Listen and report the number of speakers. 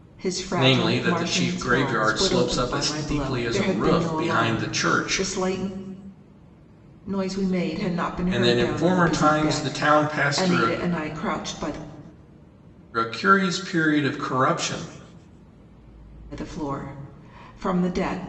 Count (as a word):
two